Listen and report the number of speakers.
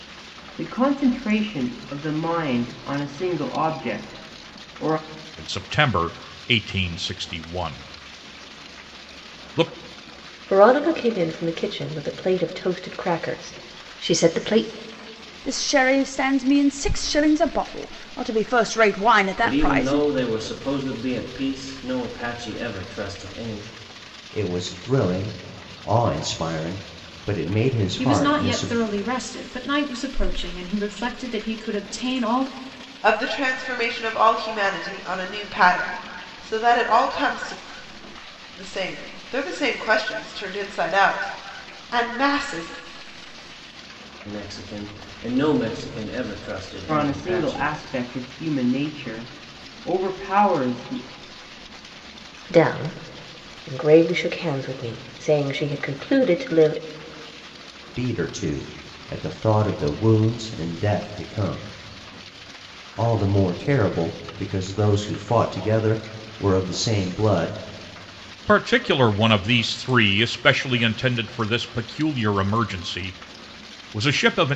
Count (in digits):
8